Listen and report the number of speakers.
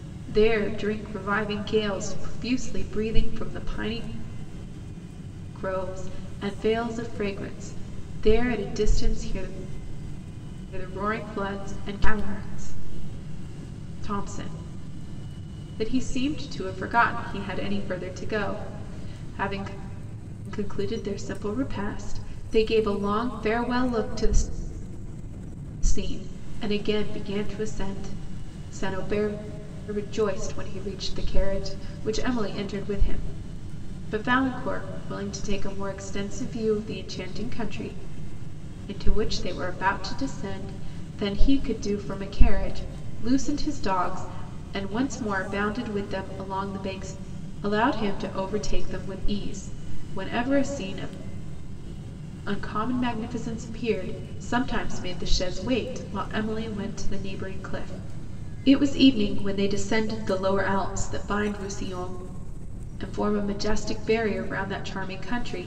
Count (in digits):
1